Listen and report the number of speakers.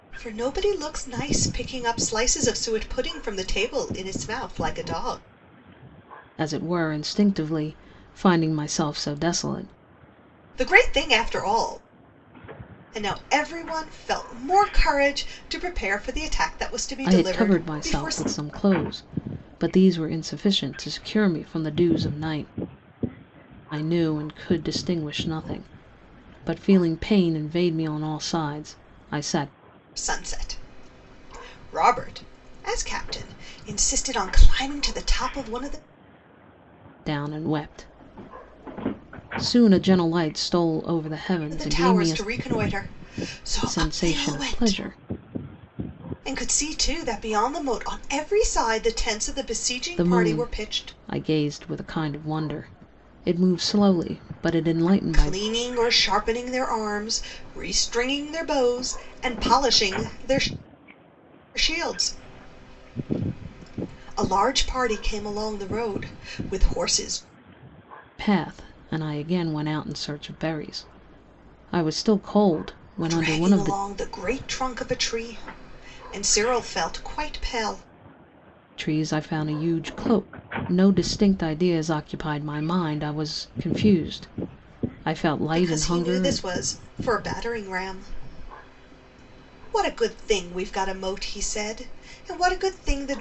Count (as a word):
two